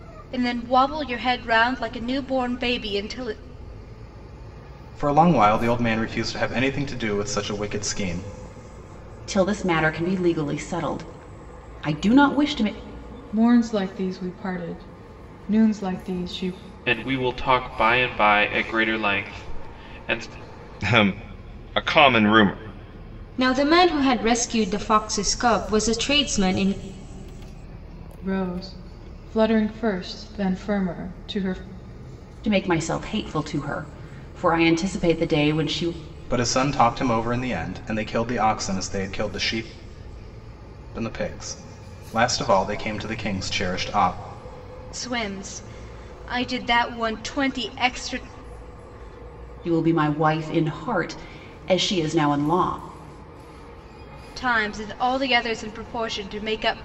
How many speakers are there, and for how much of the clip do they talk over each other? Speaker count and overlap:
7, no overlap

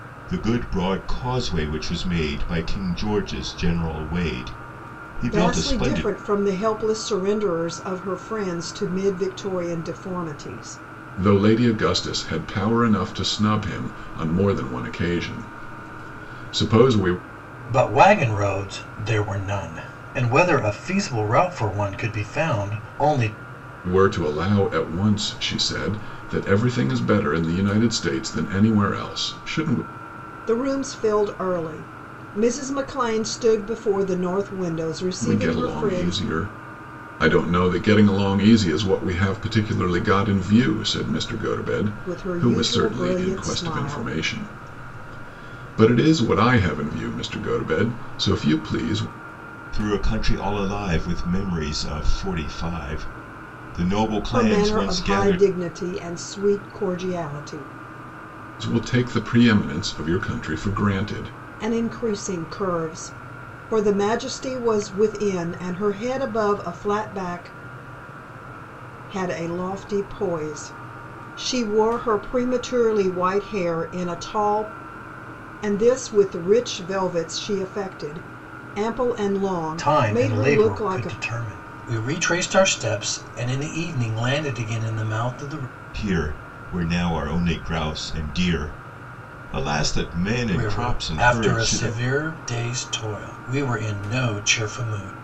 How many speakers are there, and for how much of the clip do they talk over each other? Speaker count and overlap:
4, about 9%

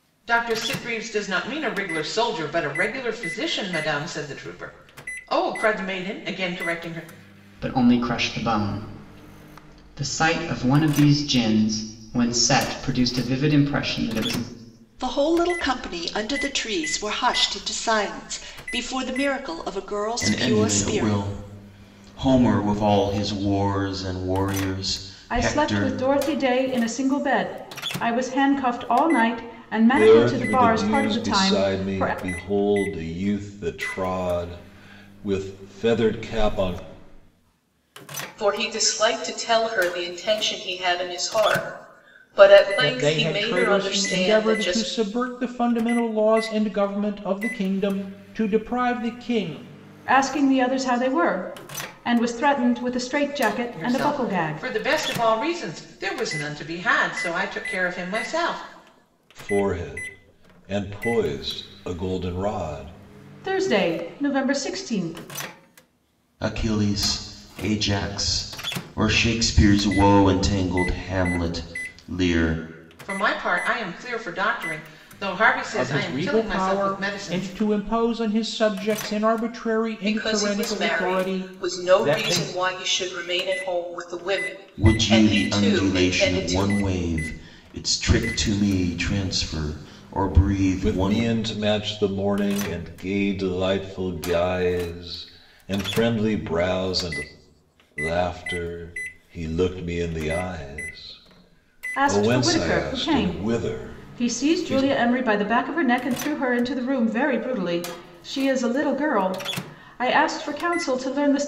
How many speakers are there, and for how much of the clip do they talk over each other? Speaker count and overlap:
8, about 15%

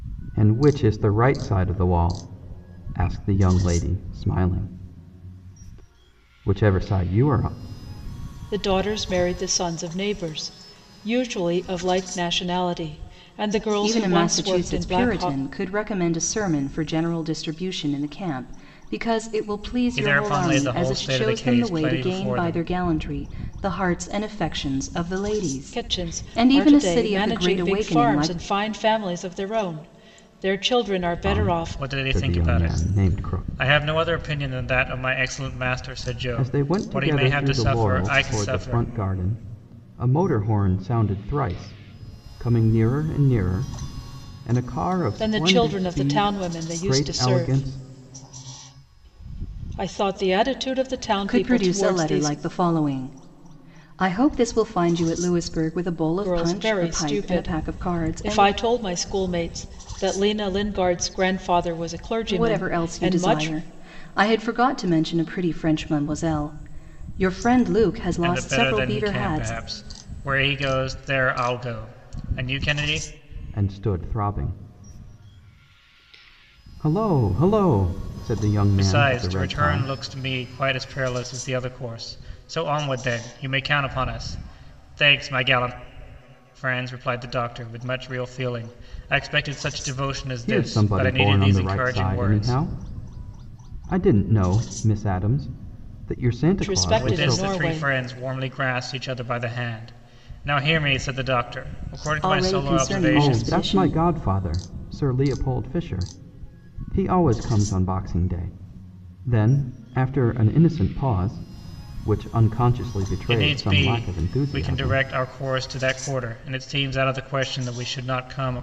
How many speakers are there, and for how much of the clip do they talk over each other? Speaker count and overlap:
4, about 25%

